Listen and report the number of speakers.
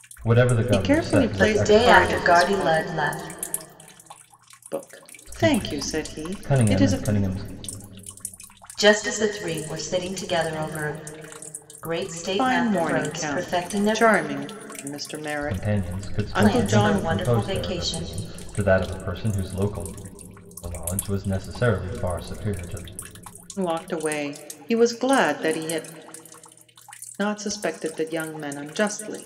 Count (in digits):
3